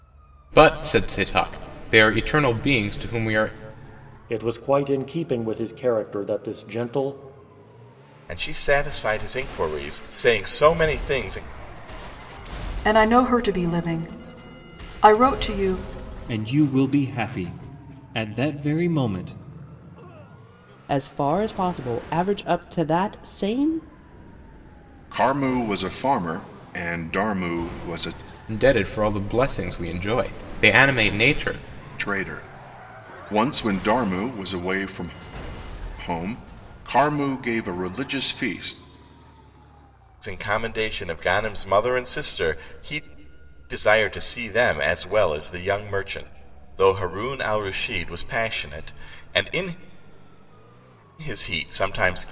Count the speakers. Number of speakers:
7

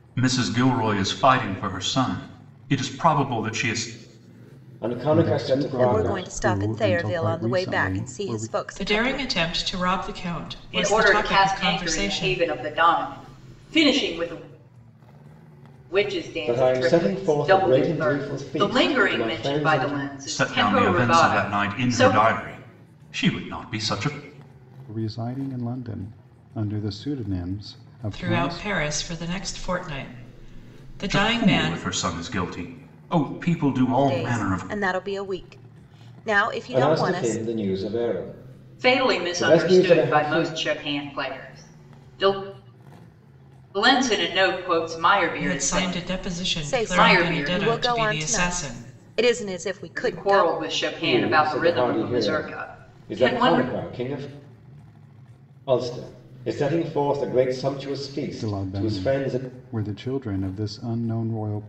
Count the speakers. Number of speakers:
6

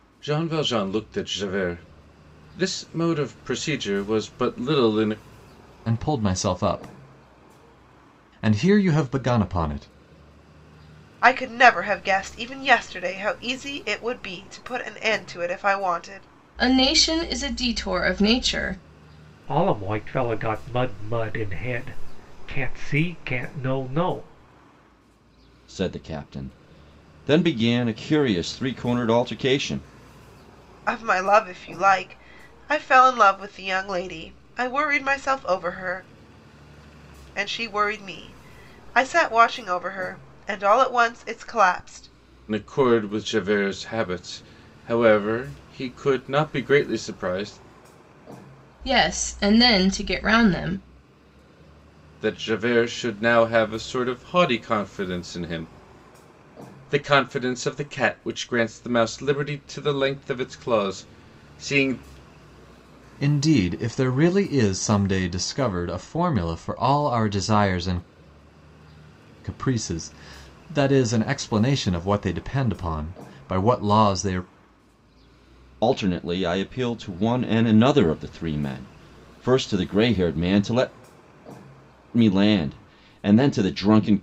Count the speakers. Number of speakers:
6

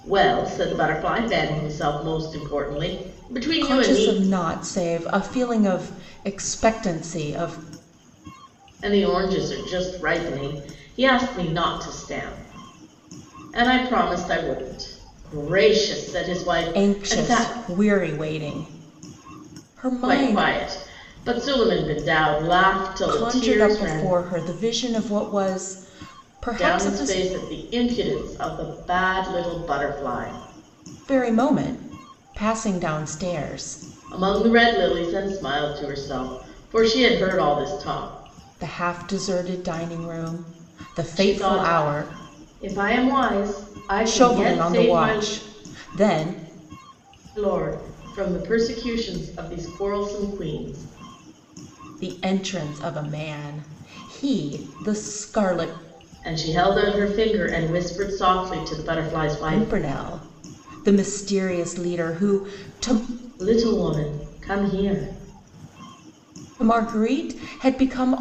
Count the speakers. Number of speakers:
2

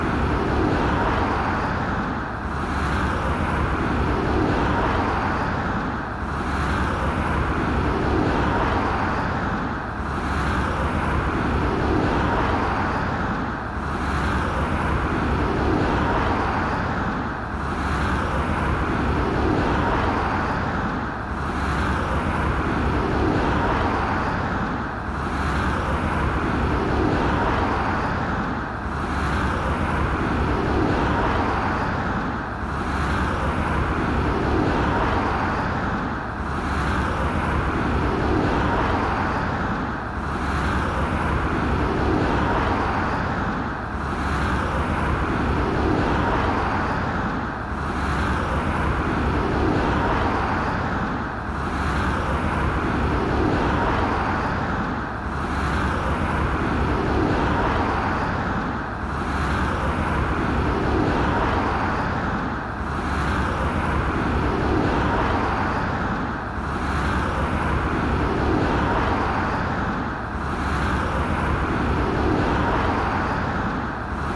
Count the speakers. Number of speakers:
0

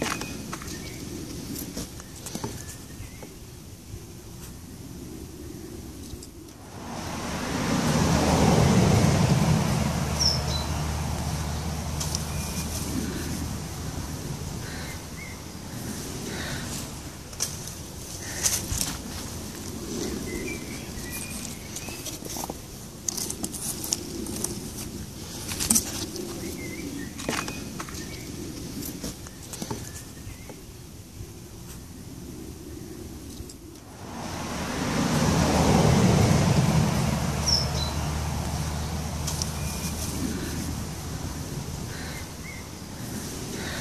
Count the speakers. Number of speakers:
0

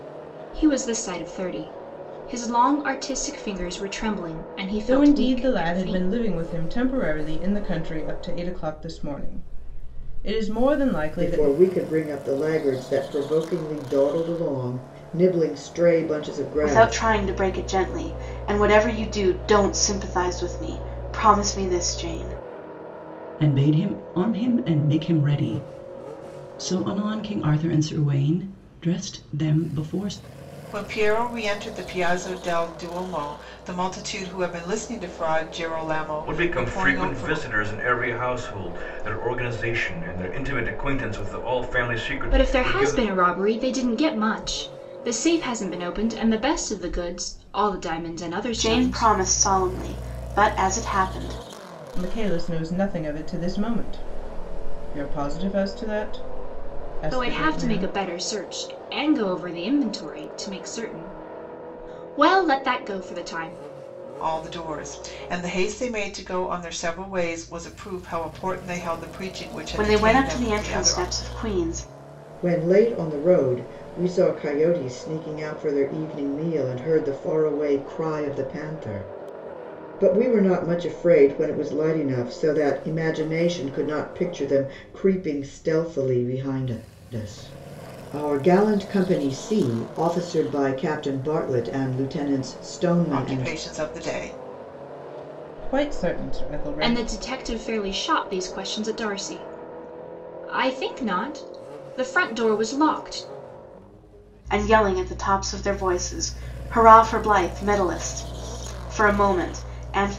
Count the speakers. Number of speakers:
7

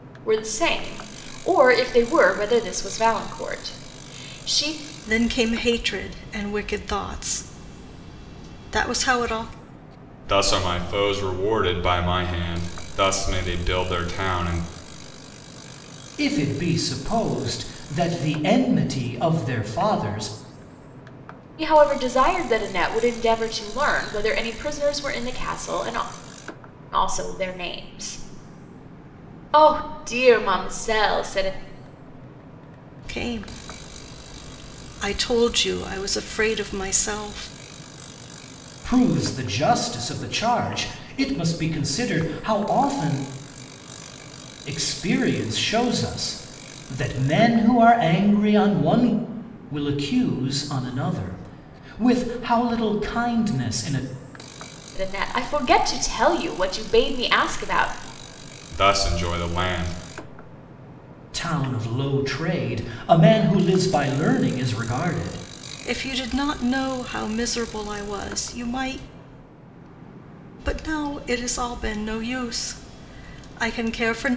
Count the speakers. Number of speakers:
4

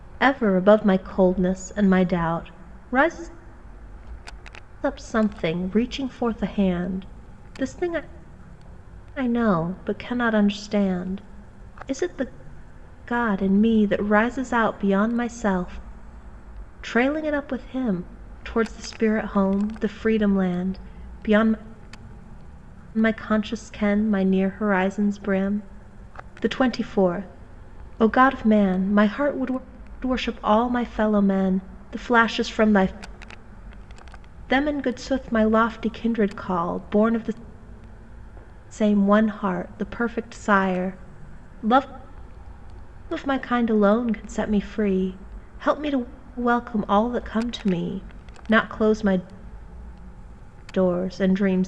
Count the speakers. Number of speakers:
1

